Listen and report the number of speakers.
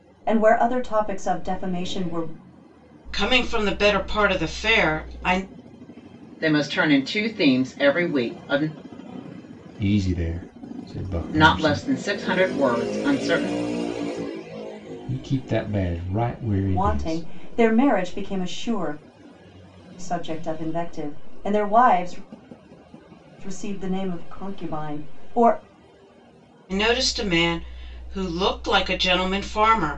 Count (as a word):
four